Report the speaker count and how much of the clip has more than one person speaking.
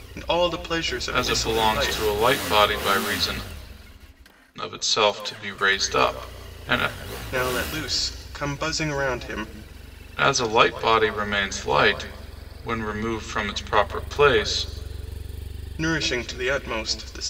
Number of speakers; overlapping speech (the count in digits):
2, about 6%